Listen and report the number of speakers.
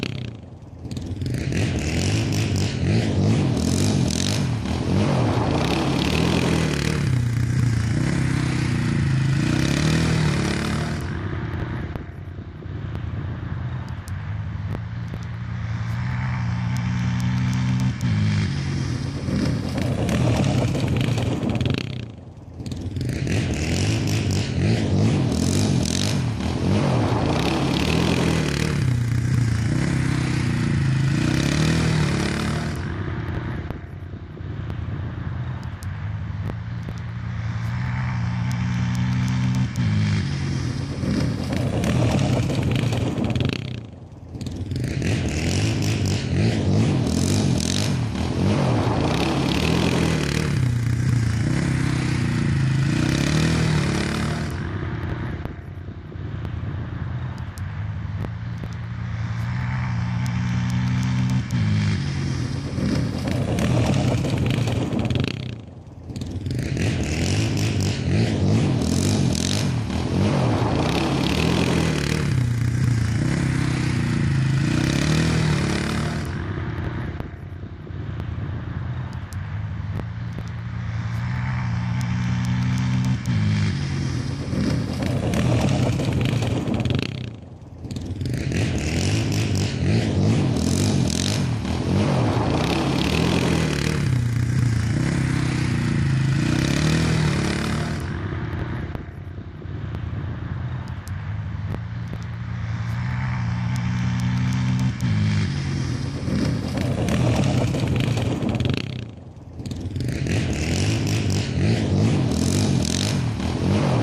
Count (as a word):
zero